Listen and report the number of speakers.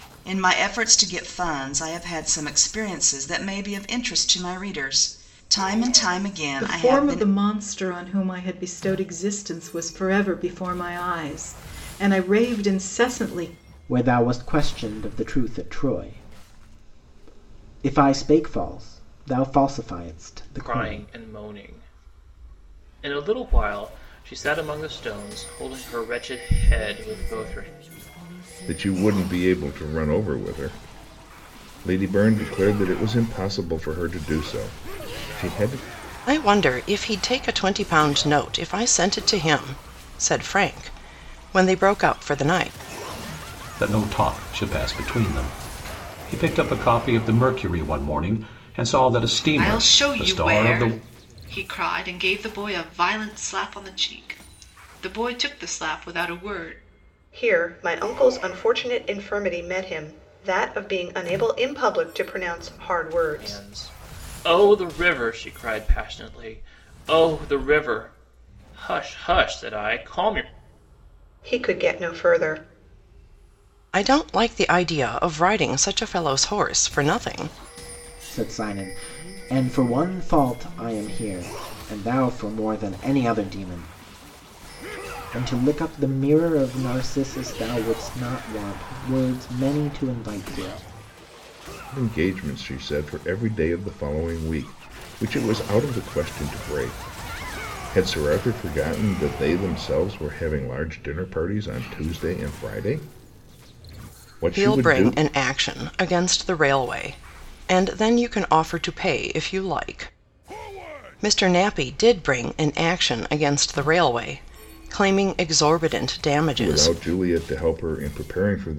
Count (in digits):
9